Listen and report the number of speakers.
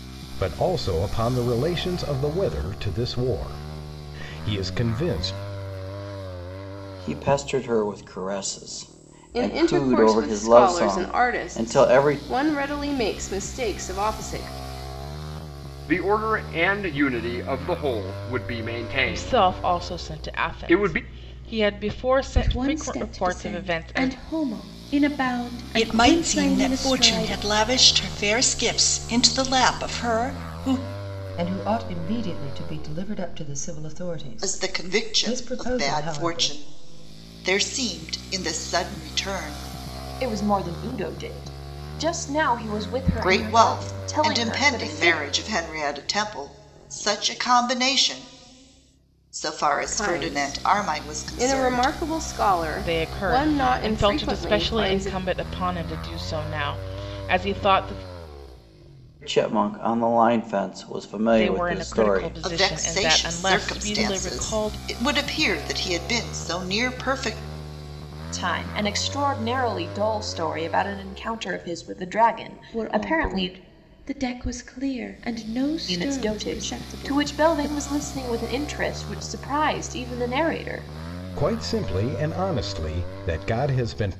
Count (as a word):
ten